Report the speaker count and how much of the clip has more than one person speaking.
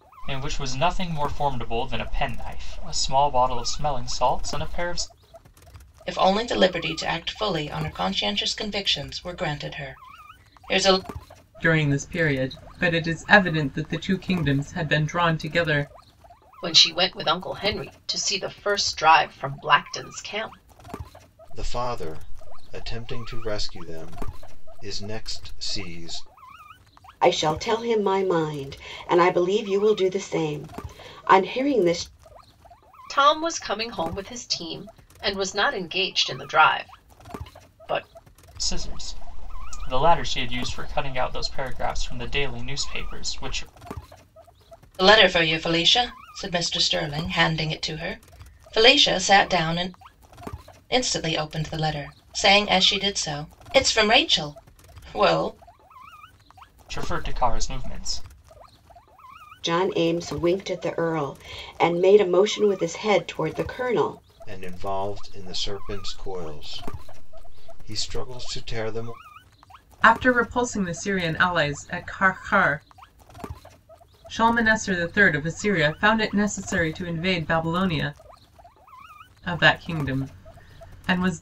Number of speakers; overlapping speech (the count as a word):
six, no overlap